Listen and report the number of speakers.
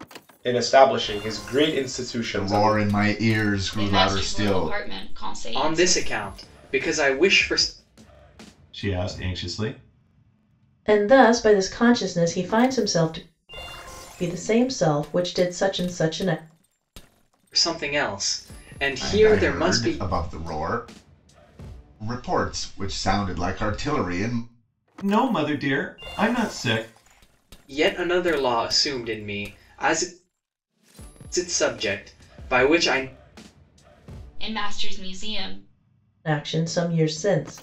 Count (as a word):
six